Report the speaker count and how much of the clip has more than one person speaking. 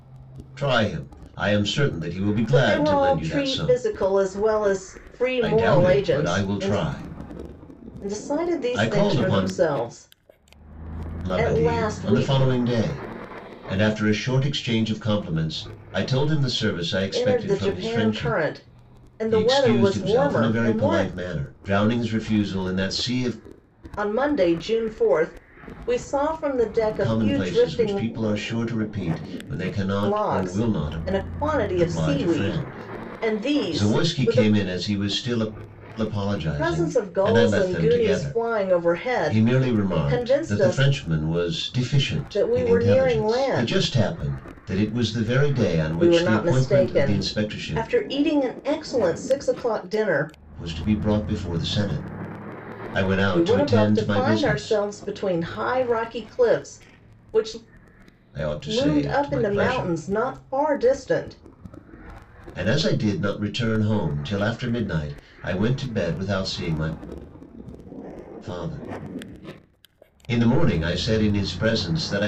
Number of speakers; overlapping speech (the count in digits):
2, about 32%